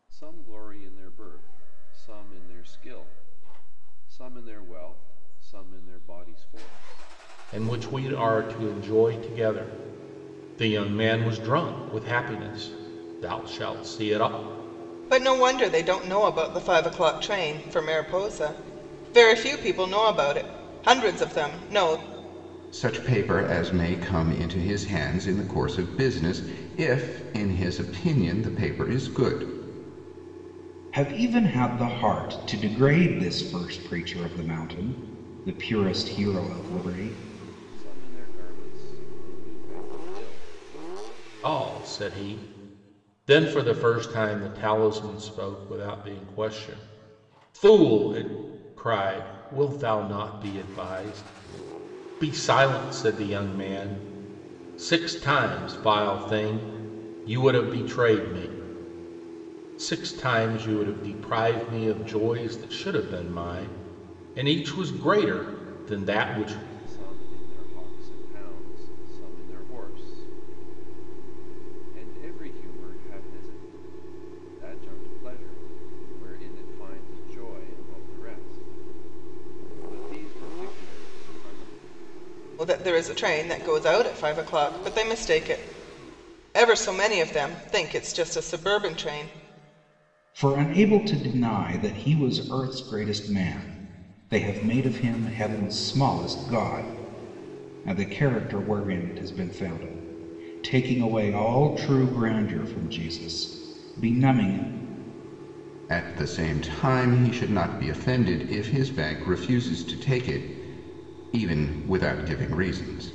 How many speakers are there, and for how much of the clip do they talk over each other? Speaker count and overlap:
five, no overlap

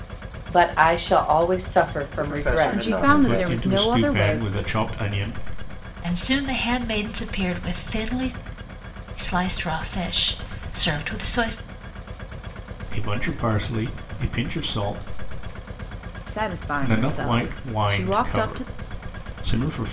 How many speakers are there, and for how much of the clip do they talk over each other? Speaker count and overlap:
five, about 22%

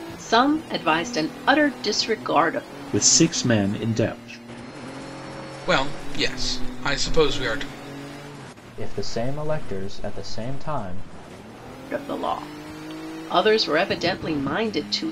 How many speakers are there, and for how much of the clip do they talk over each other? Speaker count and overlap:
four, no overlap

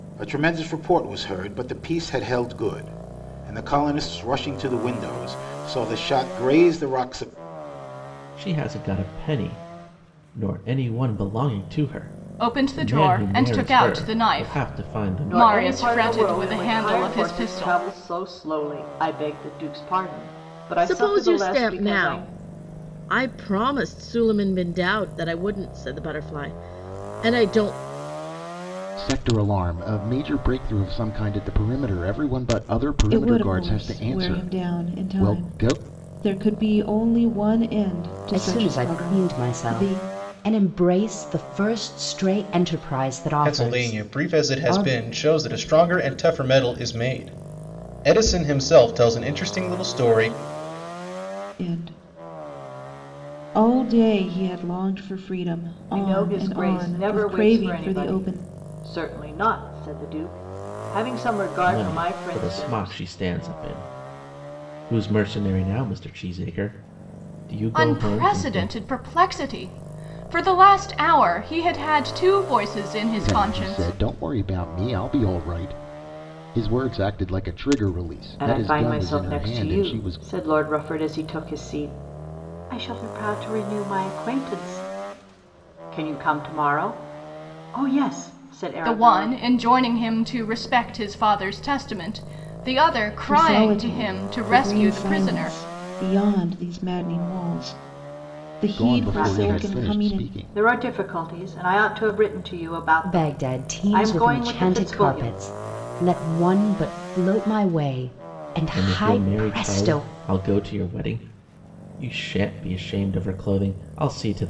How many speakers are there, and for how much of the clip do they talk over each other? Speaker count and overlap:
nine, about 25%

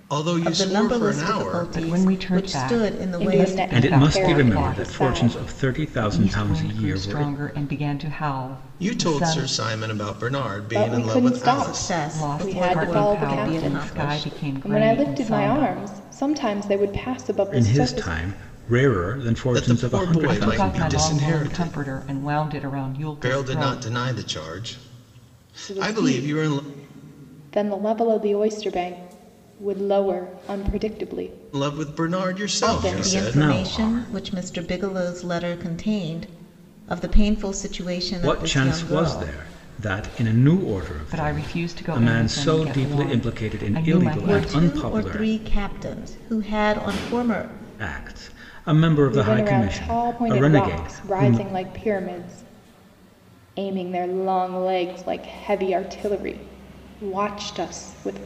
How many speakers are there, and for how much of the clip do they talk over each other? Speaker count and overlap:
five, about 46%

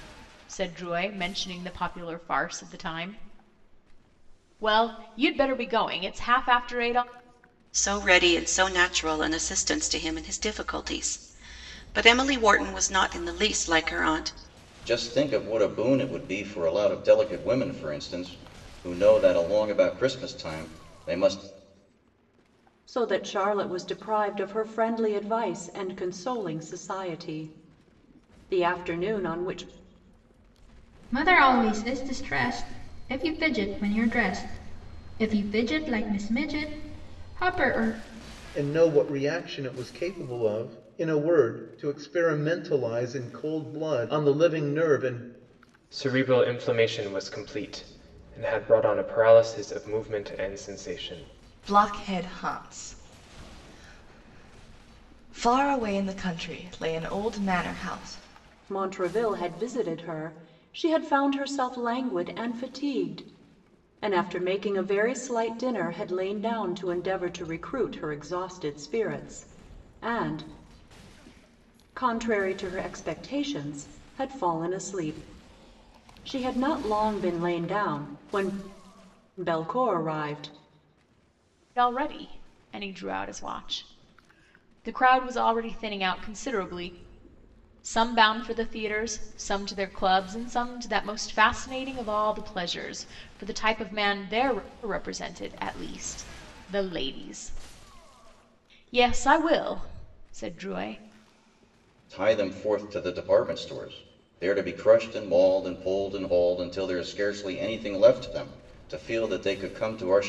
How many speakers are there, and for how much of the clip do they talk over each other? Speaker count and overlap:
eight, no overlap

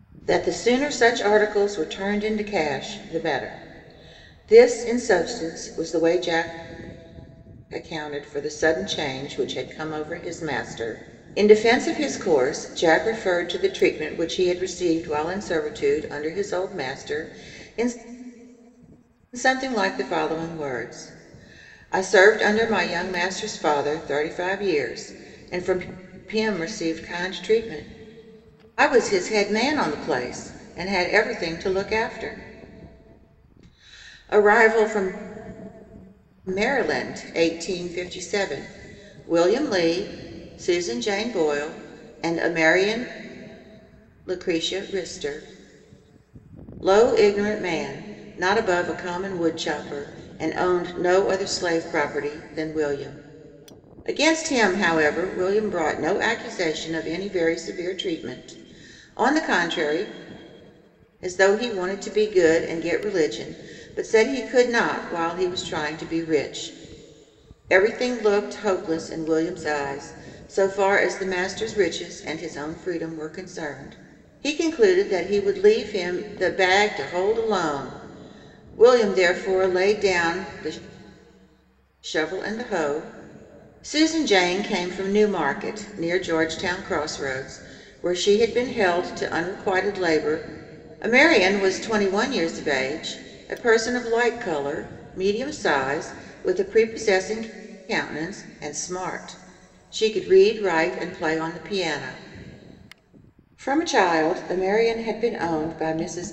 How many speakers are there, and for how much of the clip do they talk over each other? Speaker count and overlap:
one, no overlap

